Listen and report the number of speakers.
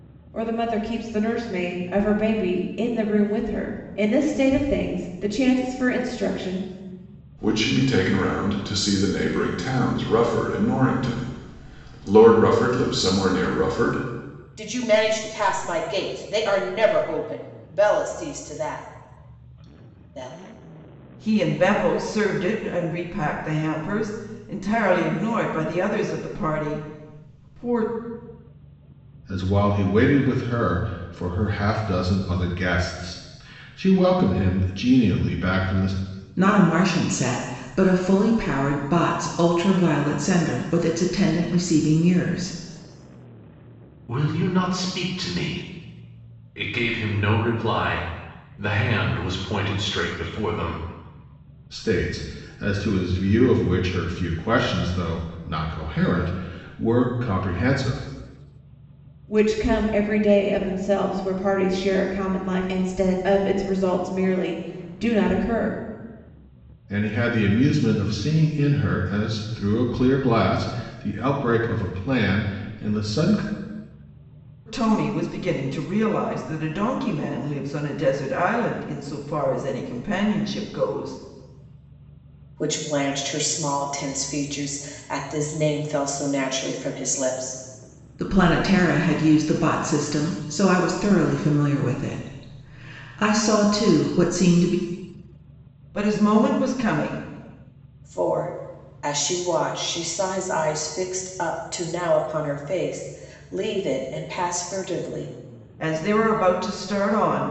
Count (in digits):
7